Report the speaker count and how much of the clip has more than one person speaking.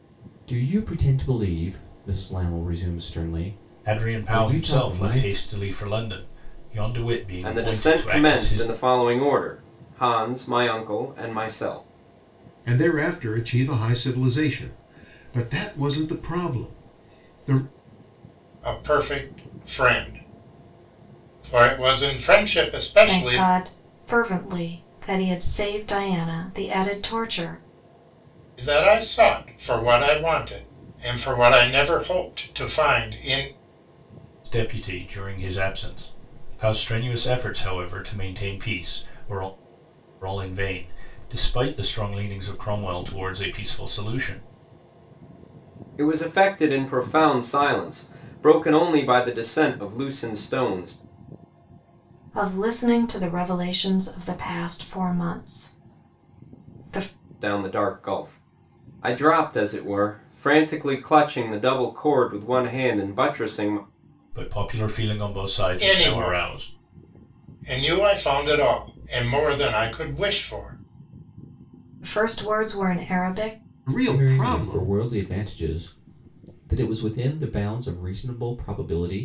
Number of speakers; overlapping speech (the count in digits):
6, about 6%